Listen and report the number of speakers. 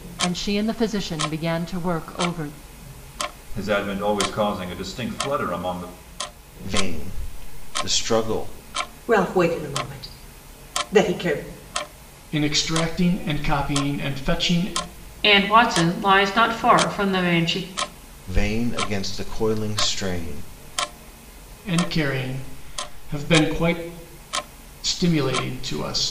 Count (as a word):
six